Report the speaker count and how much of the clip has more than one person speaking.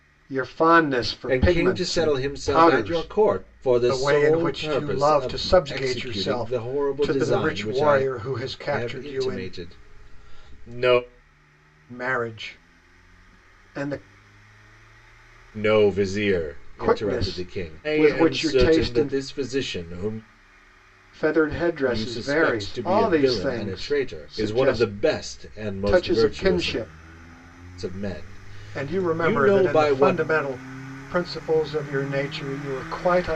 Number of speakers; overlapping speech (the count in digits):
2, about 45%